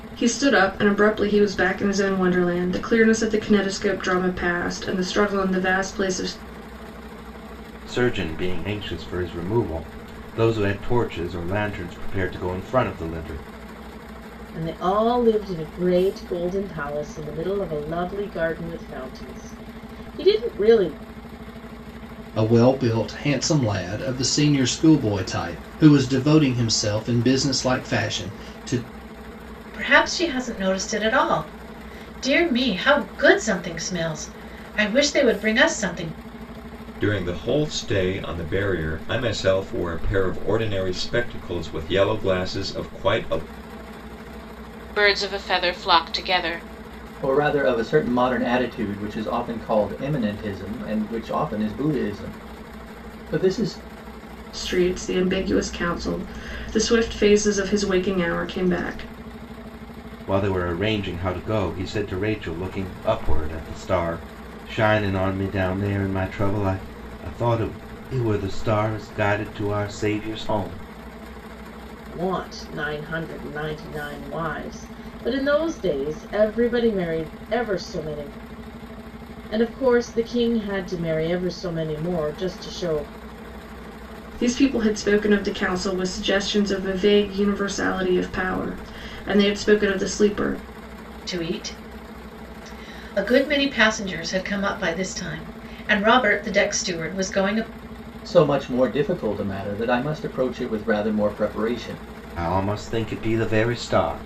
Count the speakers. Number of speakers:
8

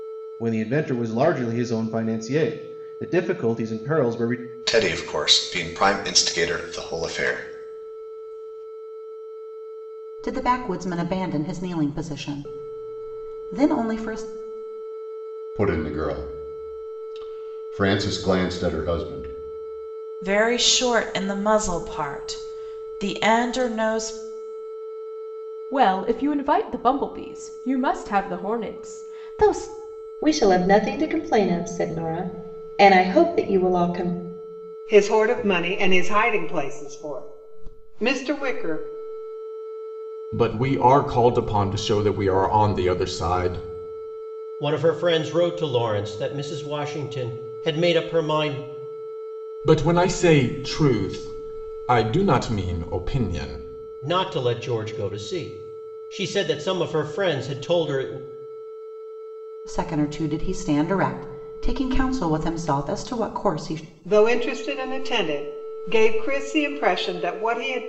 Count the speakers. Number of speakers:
10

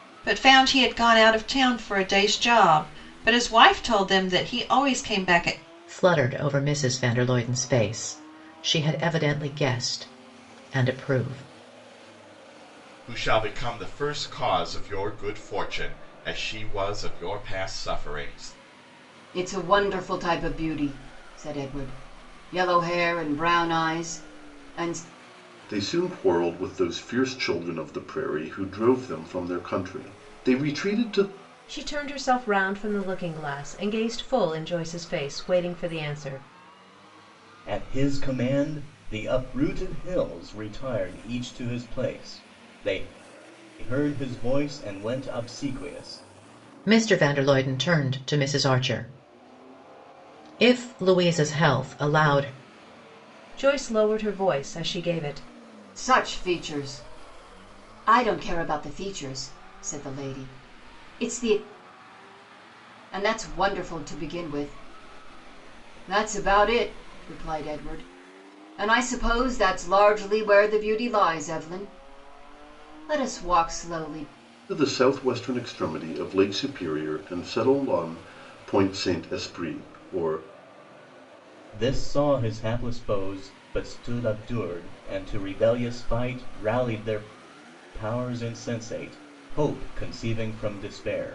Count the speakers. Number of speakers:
7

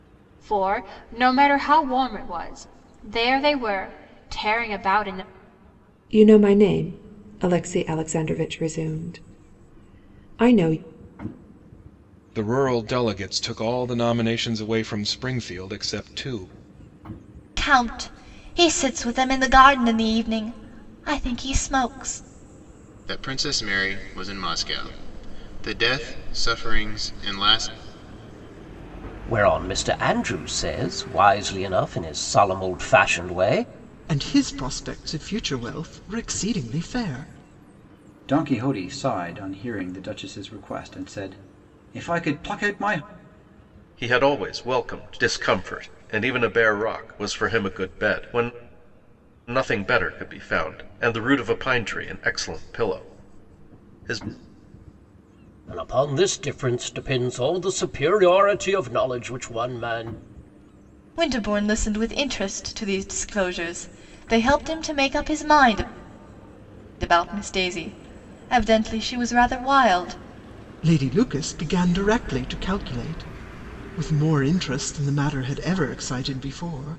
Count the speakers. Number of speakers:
9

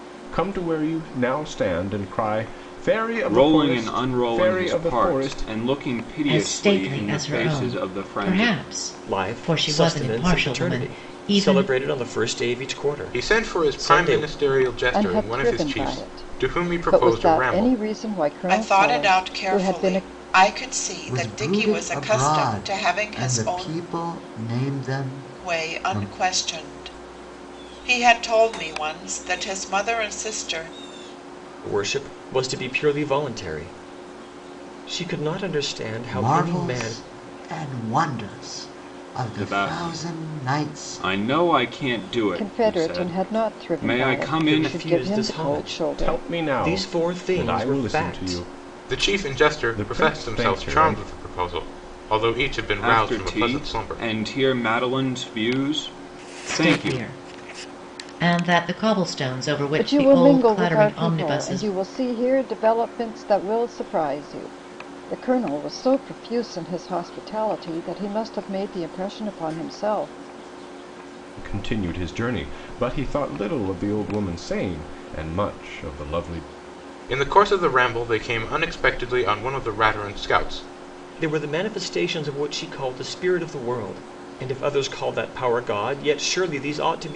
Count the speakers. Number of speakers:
8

